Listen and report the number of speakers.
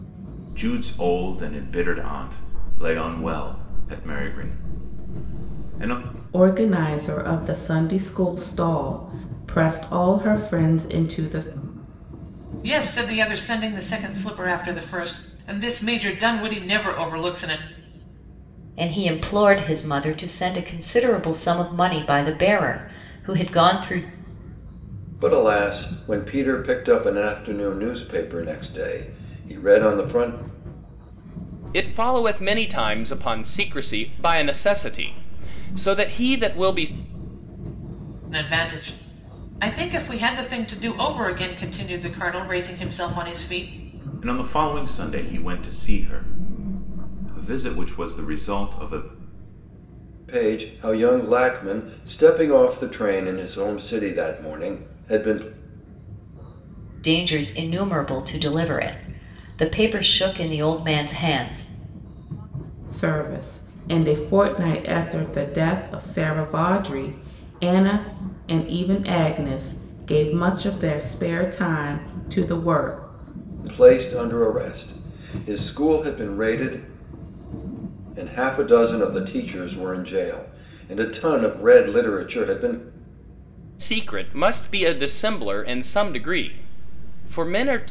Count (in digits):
6